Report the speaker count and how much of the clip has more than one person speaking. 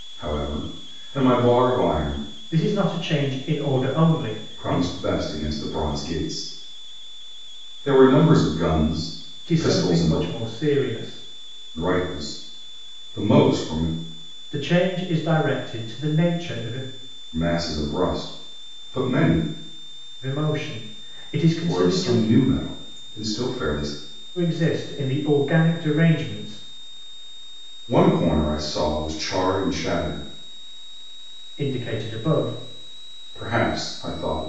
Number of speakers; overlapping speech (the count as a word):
two, about 5%